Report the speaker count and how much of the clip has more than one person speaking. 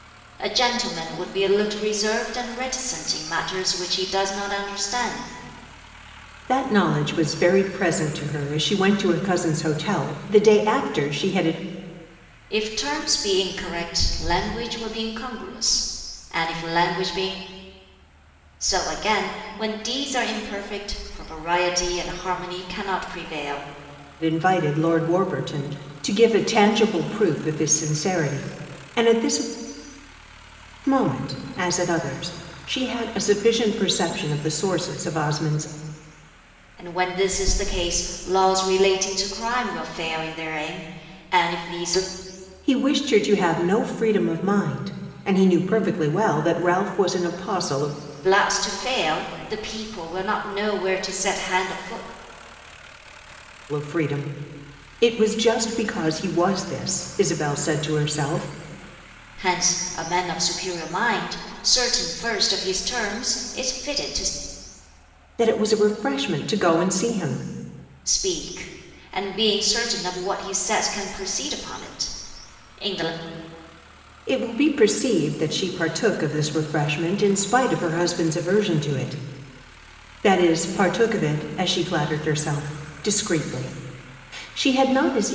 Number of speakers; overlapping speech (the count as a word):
two, no overlap